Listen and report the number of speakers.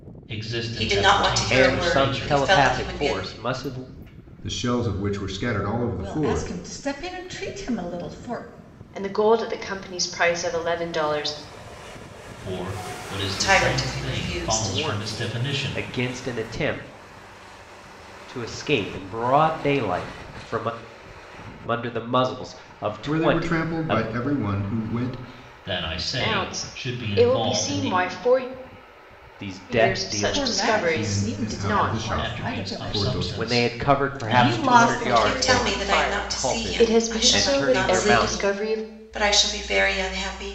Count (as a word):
six